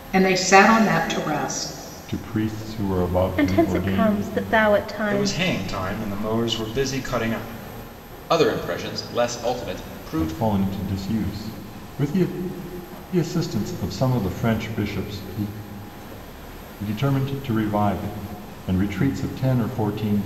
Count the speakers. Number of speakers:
5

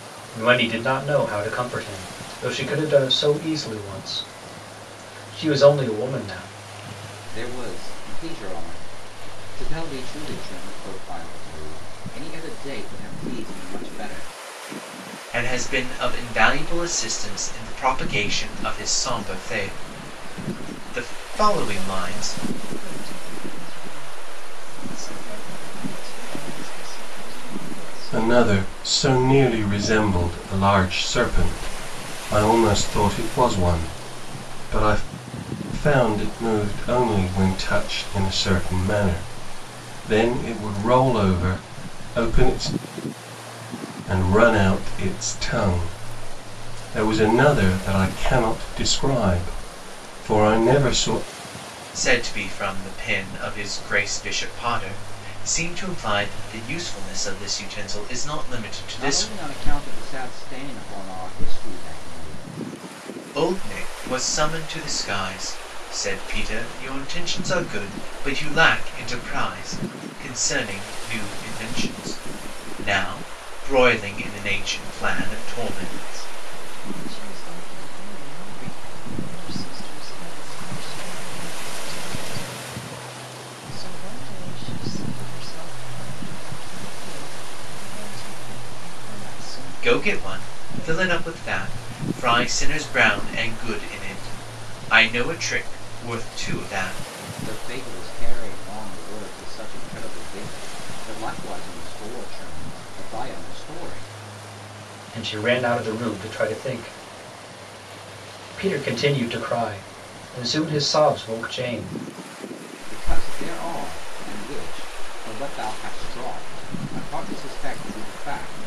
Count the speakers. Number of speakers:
5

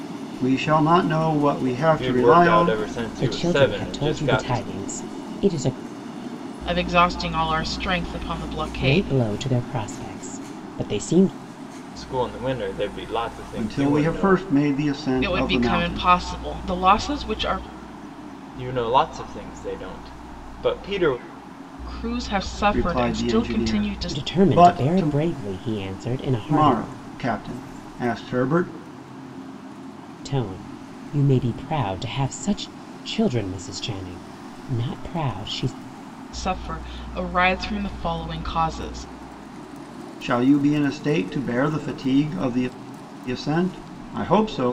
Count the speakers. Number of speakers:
4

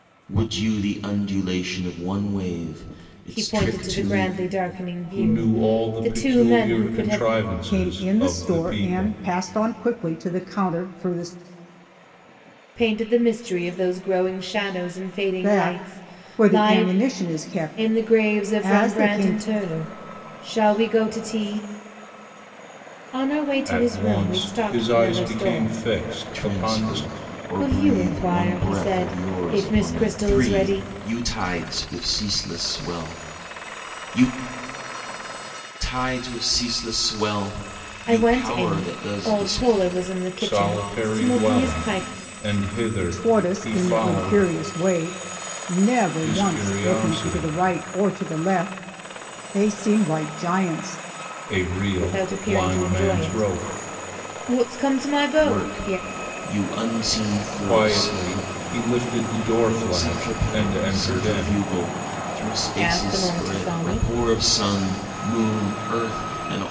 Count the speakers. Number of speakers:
4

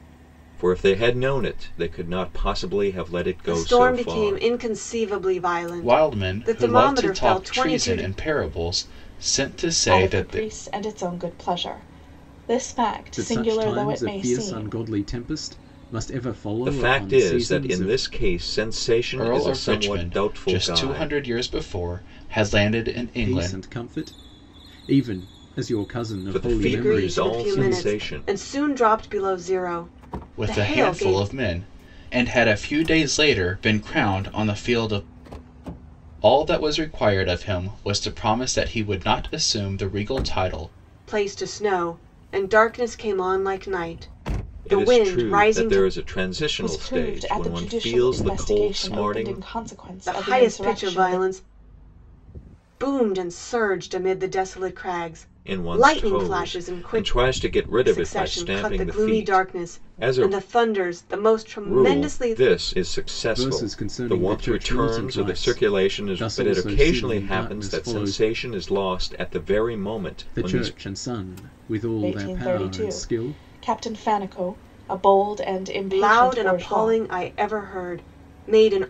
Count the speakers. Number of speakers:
5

